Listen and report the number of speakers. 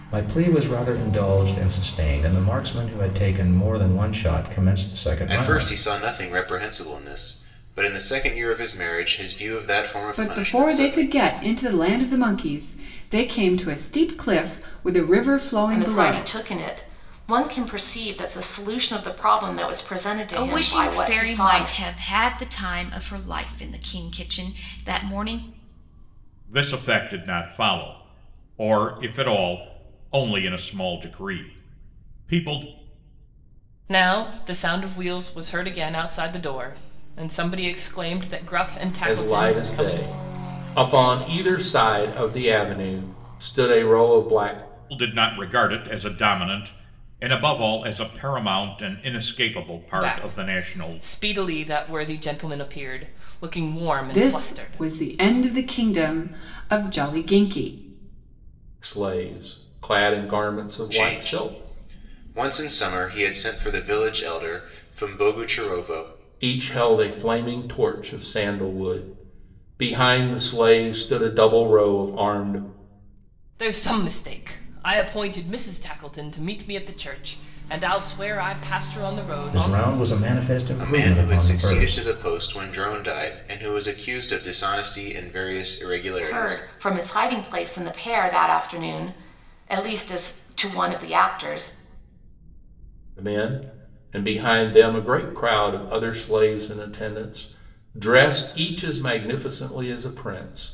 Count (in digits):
8